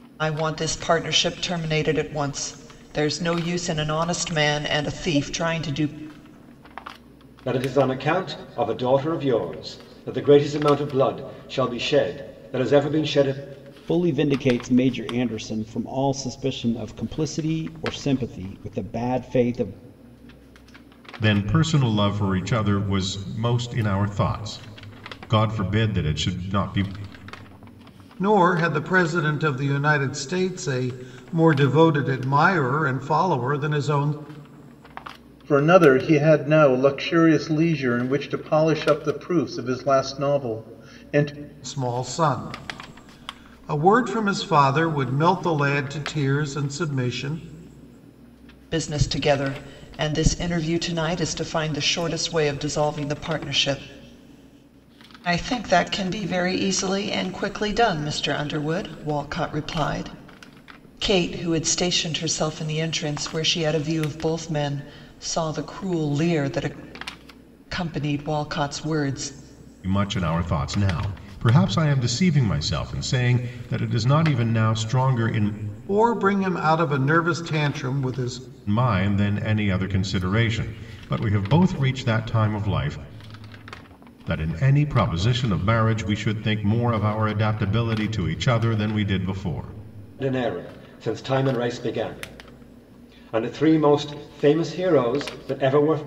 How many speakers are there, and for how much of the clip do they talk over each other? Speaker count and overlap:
6, no overlap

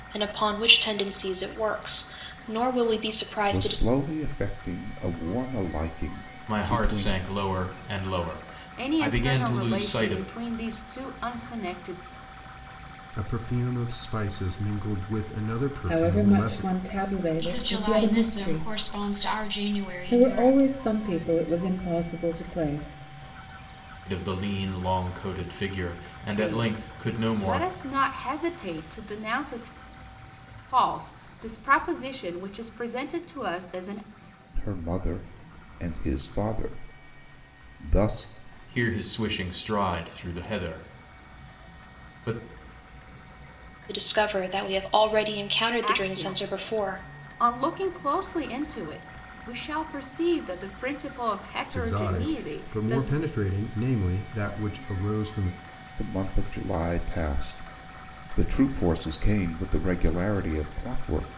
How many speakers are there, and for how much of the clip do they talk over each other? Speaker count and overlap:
7, about 16%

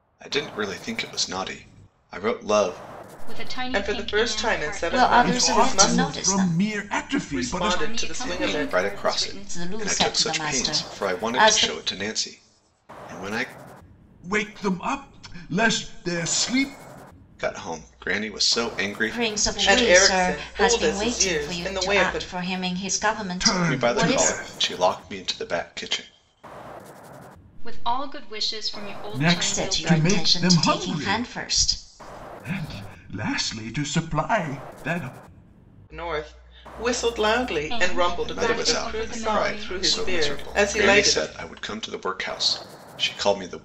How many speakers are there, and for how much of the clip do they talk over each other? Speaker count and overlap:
5, about 40%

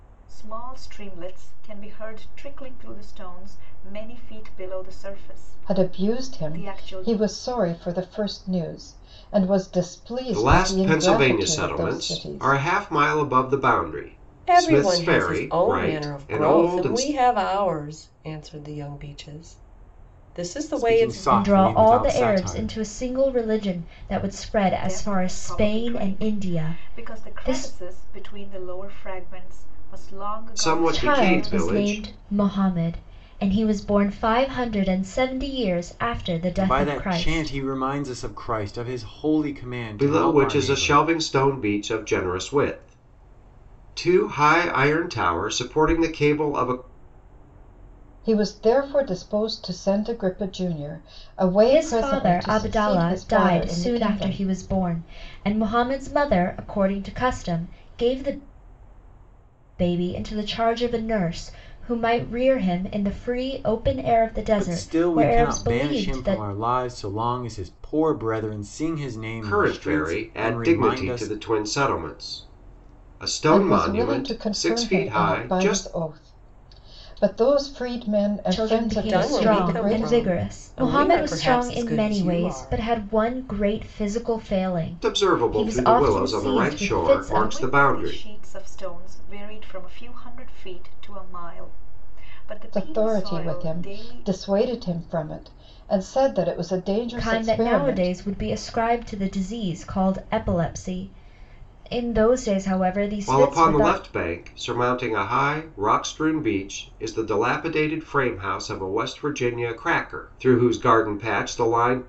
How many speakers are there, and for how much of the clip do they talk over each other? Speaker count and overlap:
6, about 32%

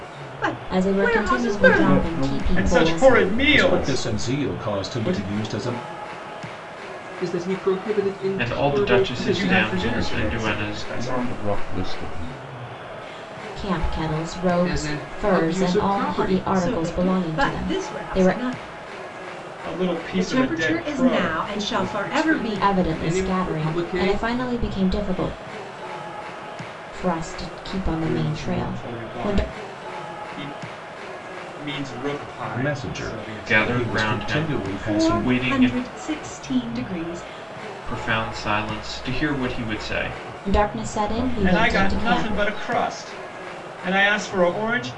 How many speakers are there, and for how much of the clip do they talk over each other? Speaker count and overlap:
7, about 48%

